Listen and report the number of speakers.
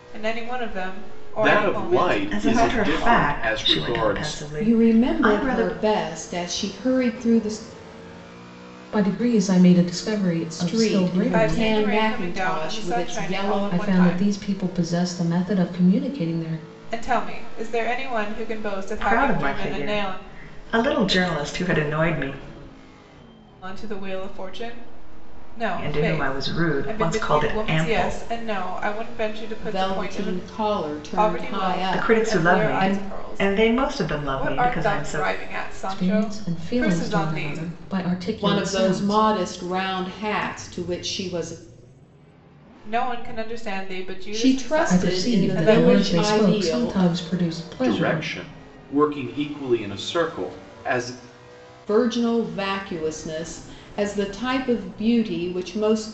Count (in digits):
5